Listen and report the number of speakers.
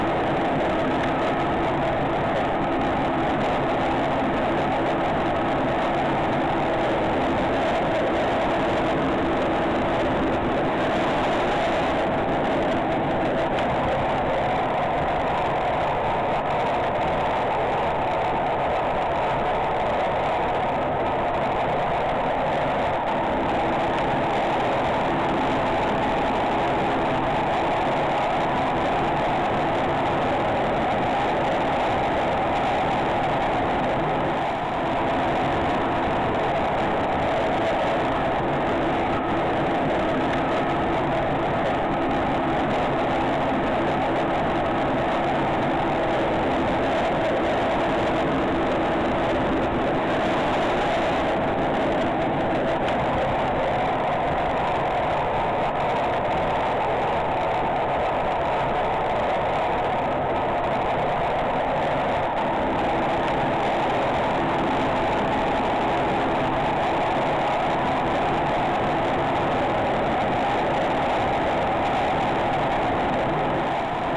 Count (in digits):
0